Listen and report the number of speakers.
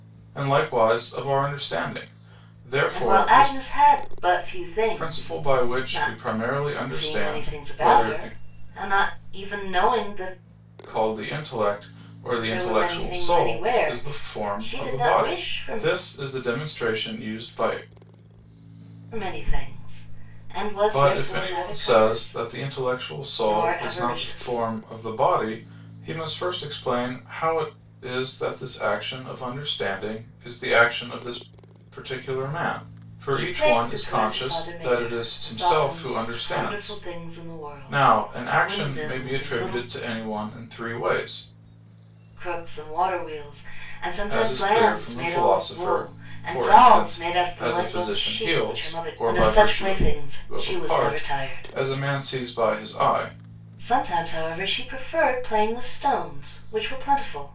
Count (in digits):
2